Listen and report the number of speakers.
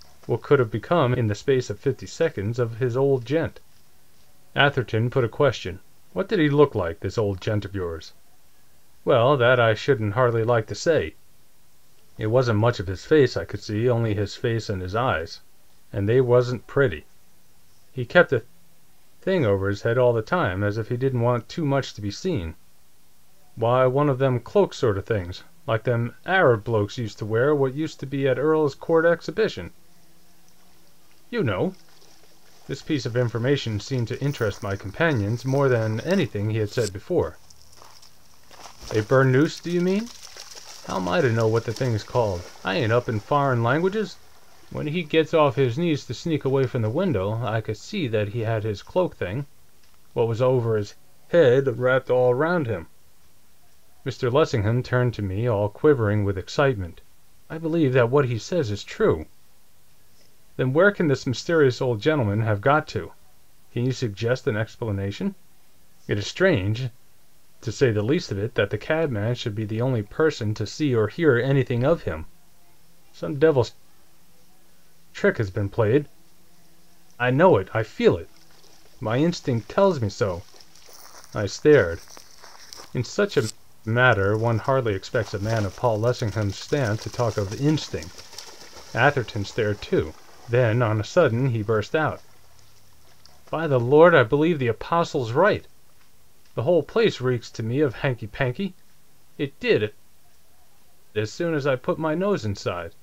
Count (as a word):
one